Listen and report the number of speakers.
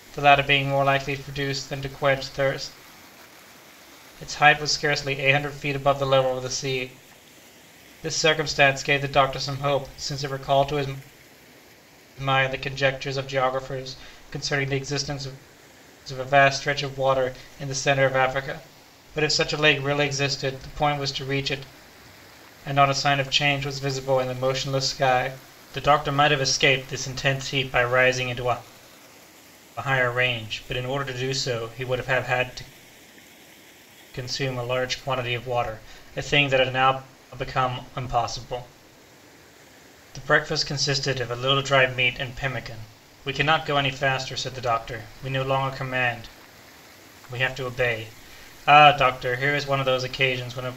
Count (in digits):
1